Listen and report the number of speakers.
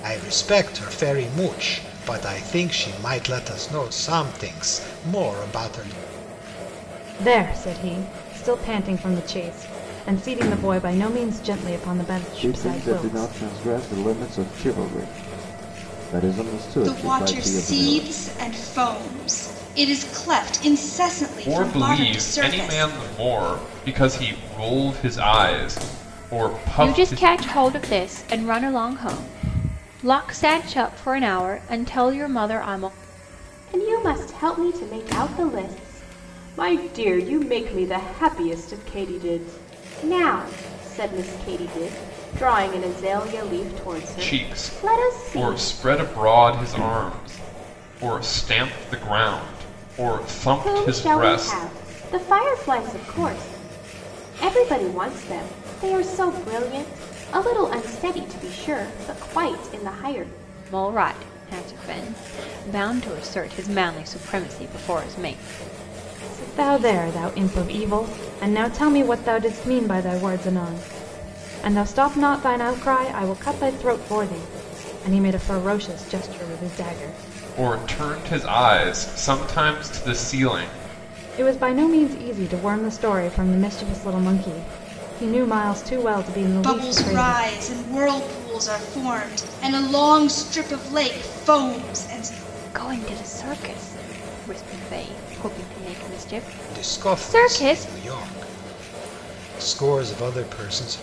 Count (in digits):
7